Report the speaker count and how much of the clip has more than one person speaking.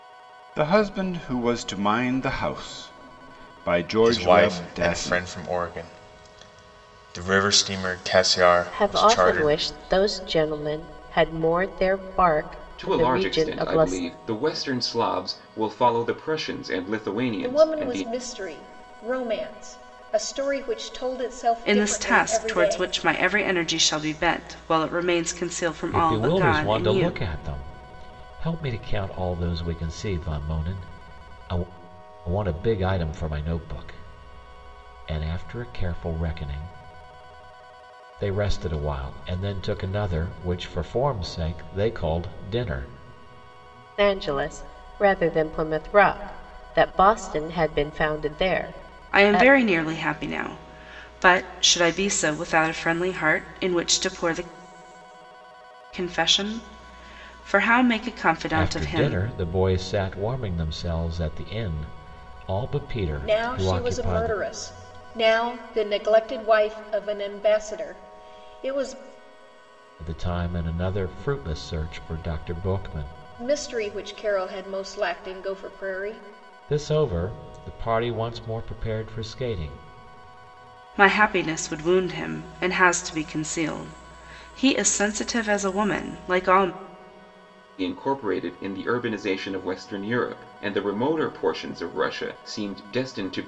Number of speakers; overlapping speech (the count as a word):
seven, about 10%